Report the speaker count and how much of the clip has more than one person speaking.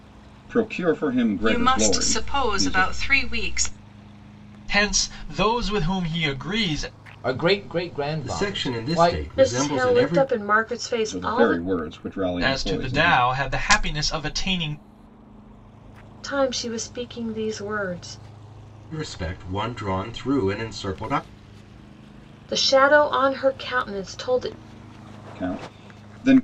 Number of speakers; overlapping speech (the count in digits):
6, about 19%